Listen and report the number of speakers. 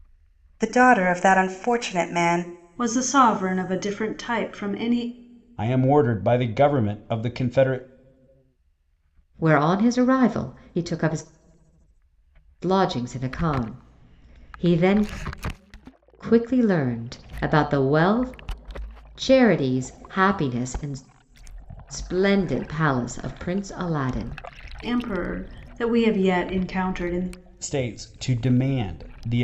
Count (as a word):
four